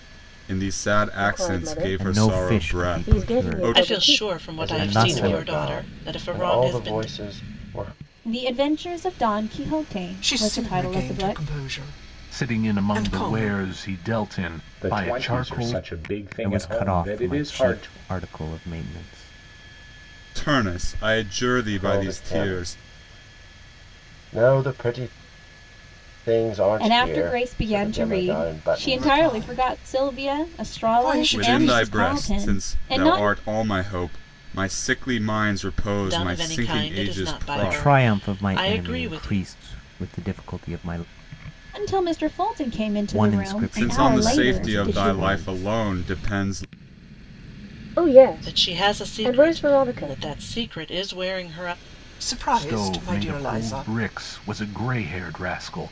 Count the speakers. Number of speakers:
9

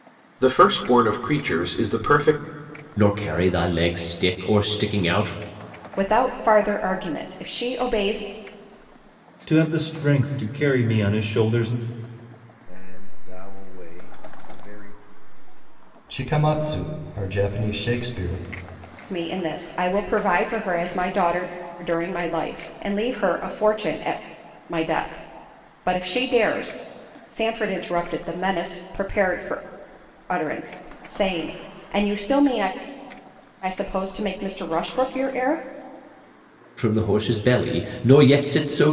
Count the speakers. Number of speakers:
6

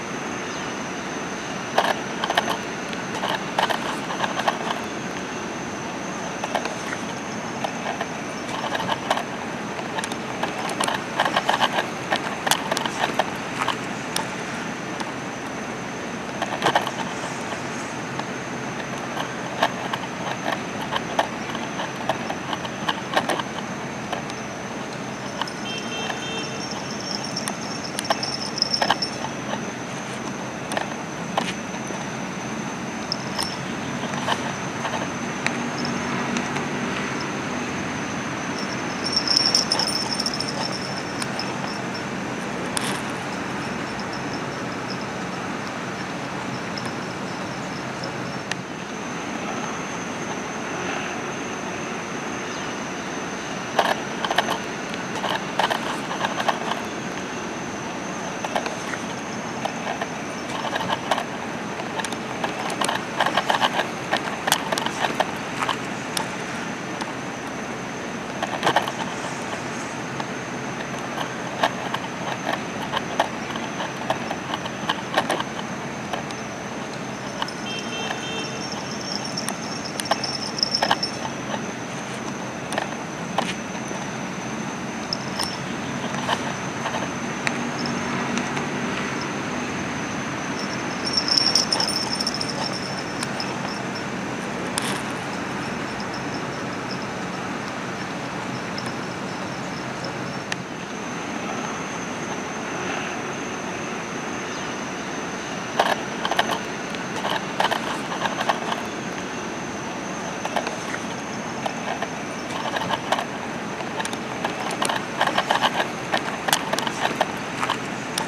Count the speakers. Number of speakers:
0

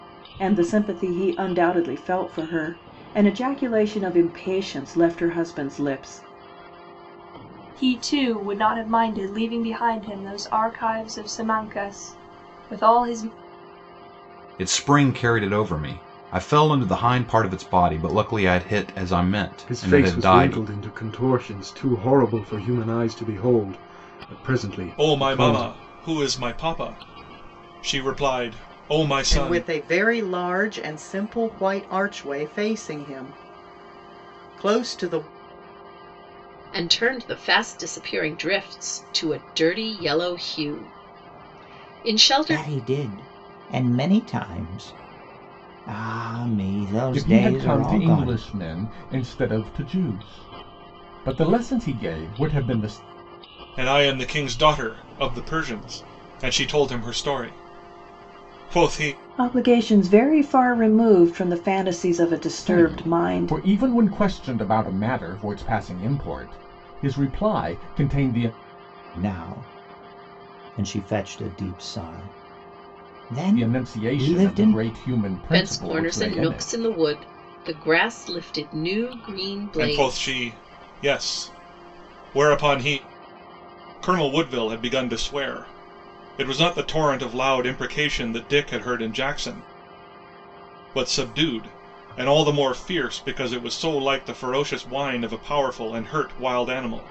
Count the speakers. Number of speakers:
9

